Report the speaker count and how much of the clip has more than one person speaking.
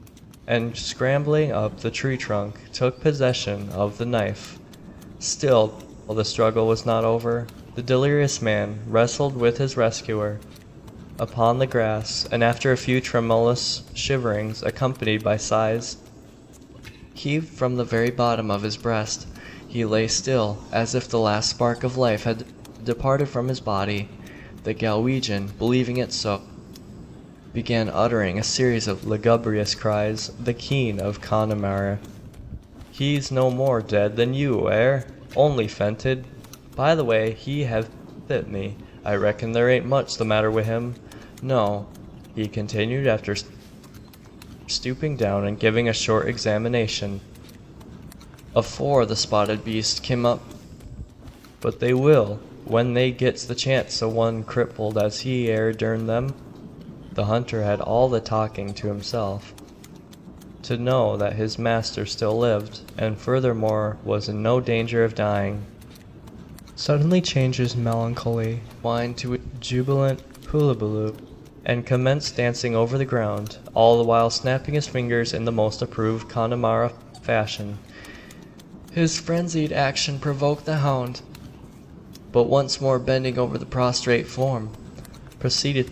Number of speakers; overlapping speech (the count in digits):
1, no overlap